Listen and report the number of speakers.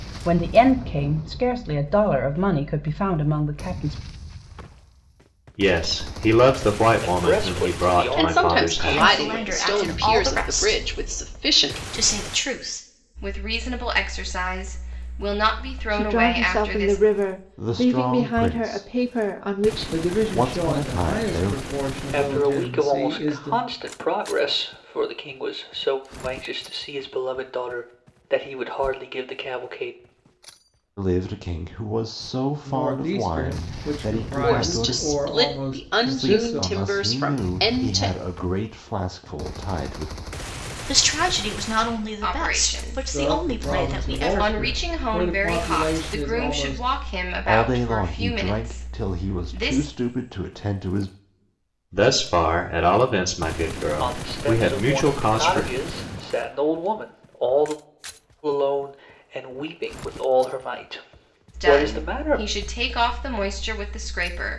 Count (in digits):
9